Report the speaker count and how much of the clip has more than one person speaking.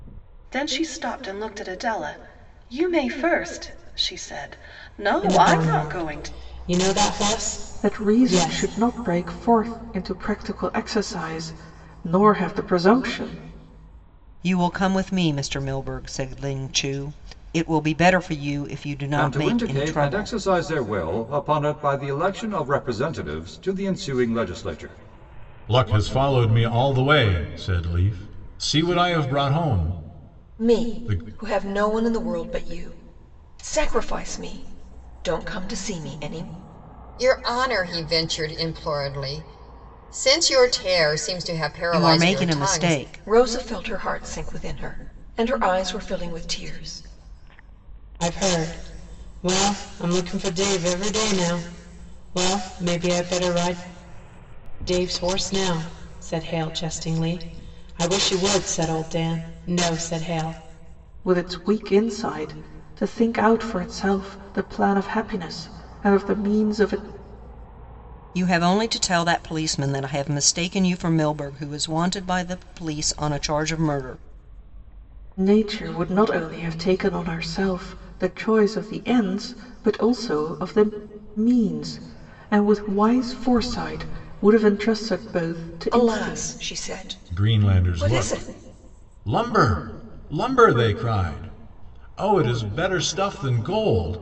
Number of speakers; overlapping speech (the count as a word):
eight, about 8%